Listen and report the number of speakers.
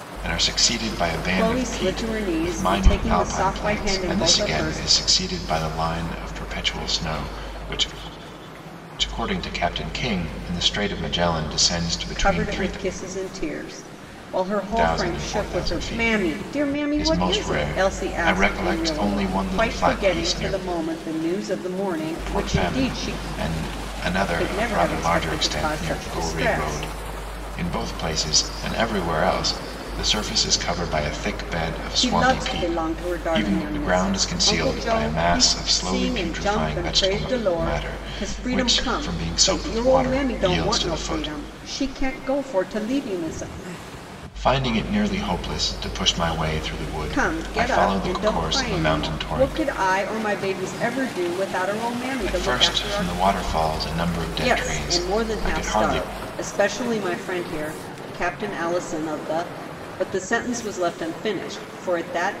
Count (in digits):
2